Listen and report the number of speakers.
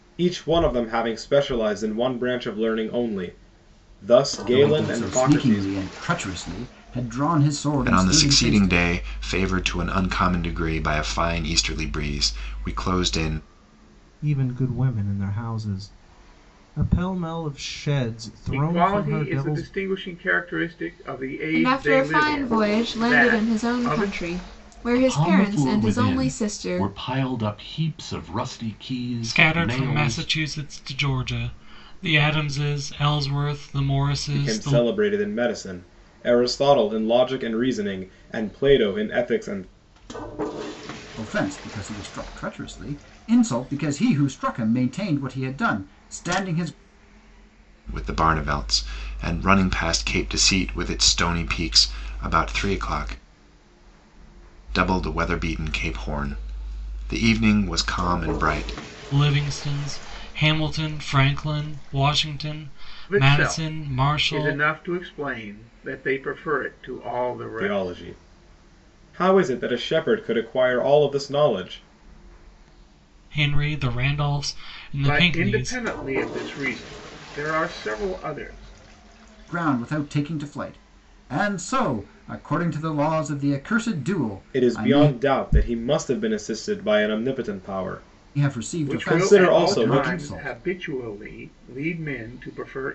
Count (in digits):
8